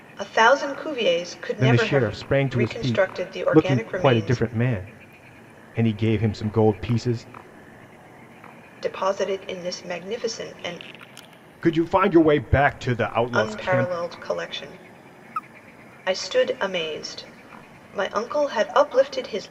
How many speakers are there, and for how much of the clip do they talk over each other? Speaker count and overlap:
two, about 17%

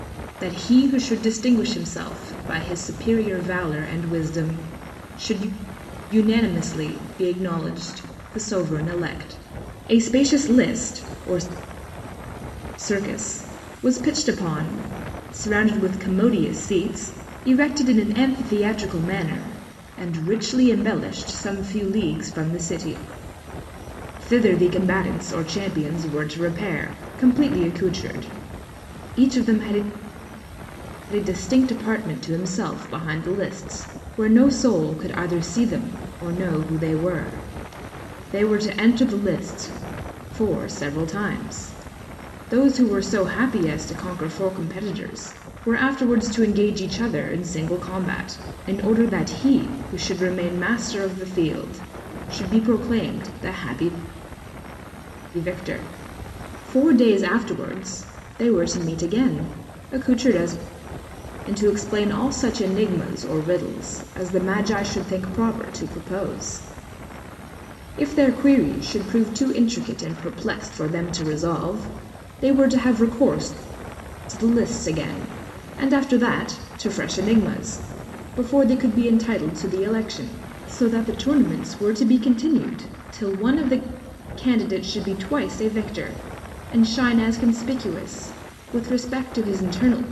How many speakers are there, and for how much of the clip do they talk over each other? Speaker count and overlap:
one, no overlap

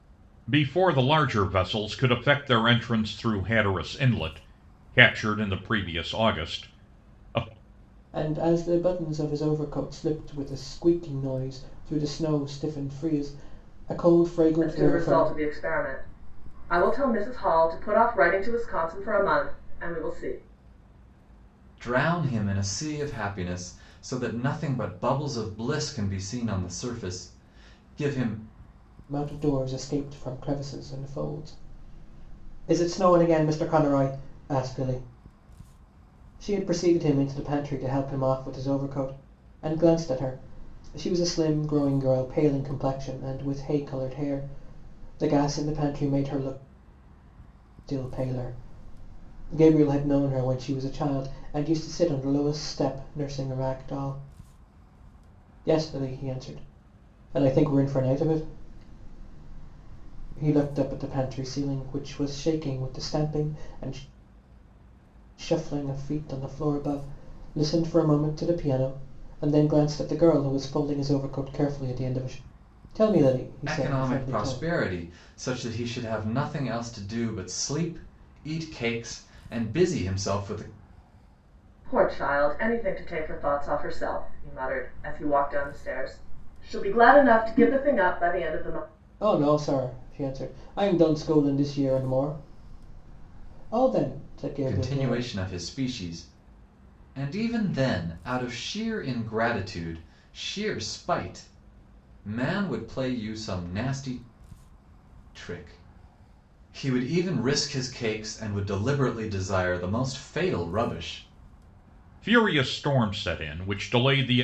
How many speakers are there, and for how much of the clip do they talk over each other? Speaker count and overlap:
four, about 2%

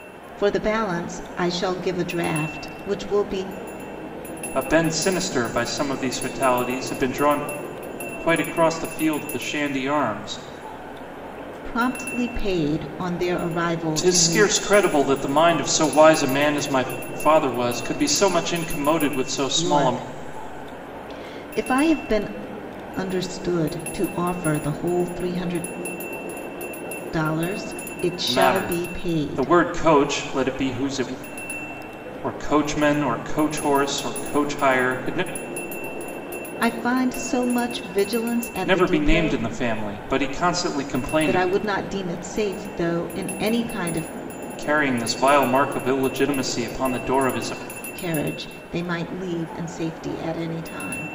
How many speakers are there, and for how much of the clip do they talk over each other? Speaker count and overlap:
two, about 7%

